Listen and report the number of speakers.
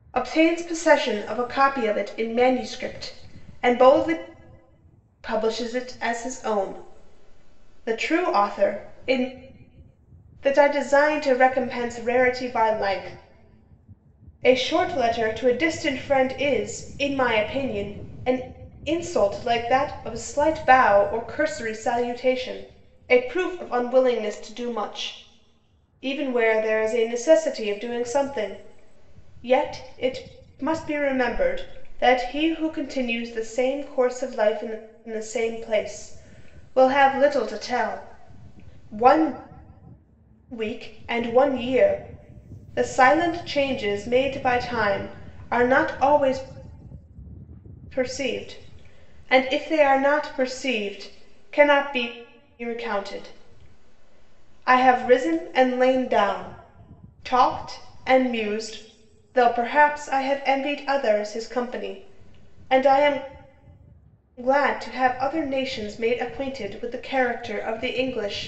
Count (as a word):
one